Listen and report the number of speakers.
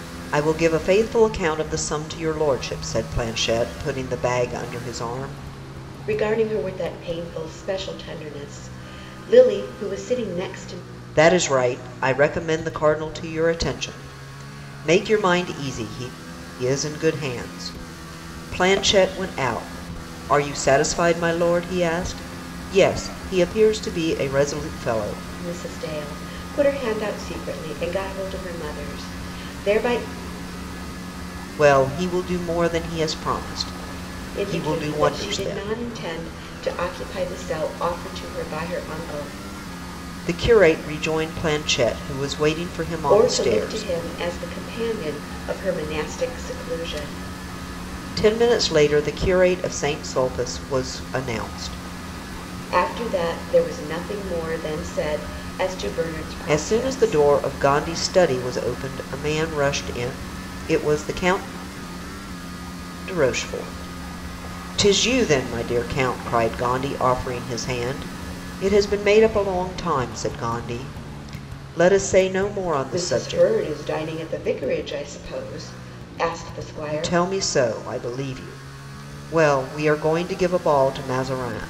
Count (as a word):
two